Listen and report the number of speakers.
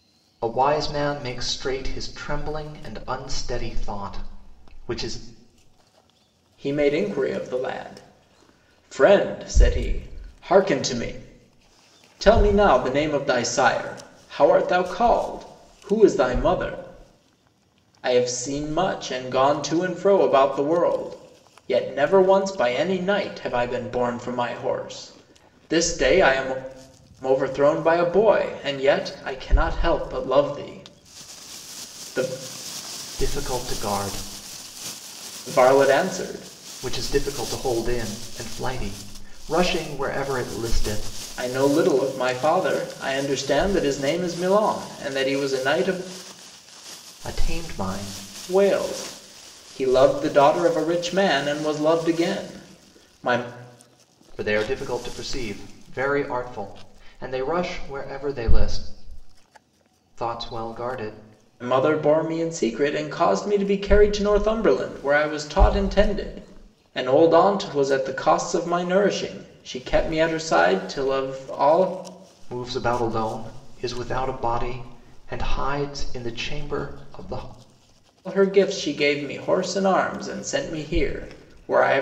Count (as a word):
two